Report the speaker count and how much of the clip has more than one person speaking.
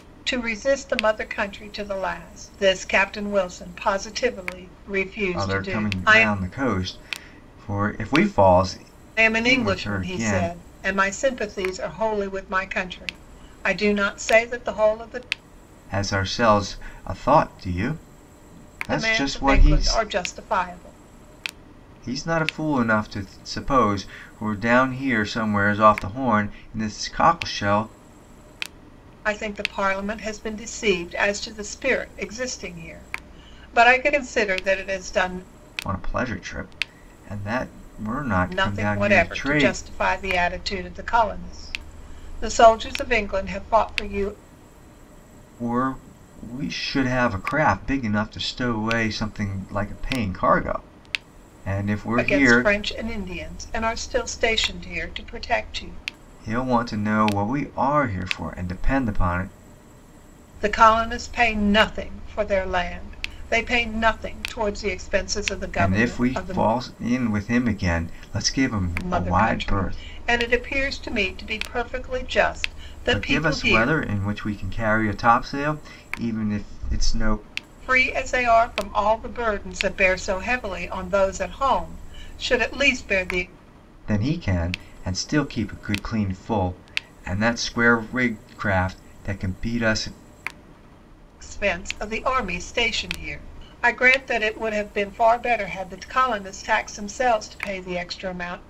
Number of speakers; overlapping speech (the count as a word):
two, about 8%